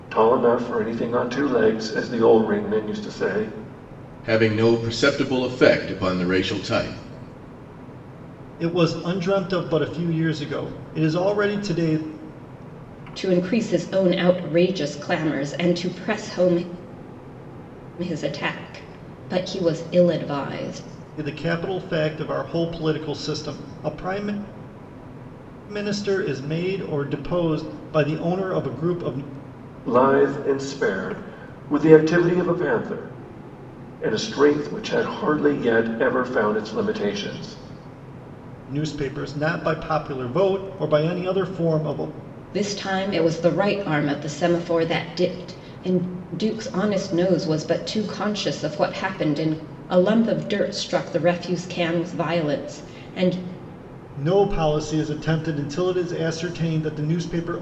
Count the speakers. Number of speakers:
4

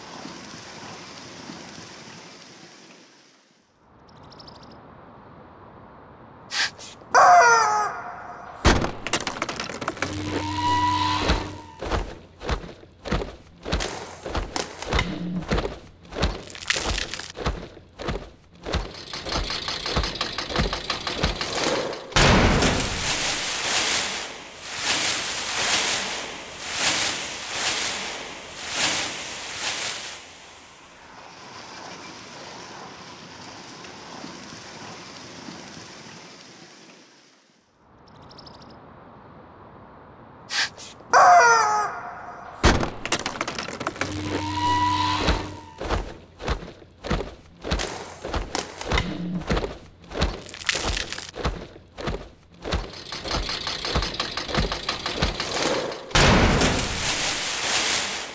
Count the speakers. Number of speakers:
0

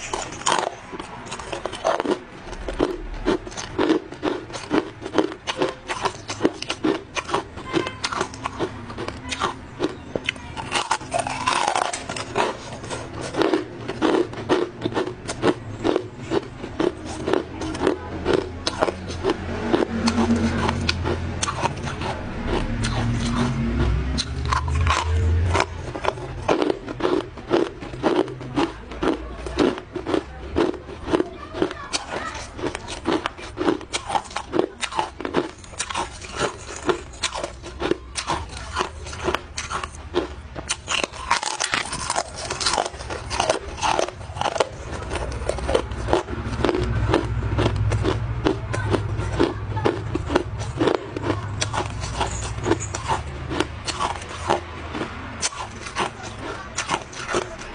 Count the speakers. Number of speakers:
0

